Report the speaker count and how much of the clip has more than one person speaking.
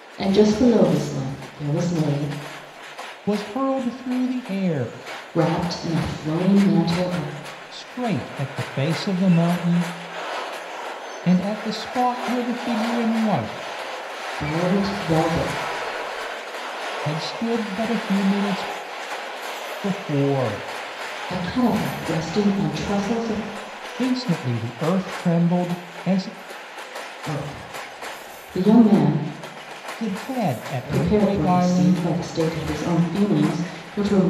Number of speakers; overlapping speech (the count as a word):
two, about 4%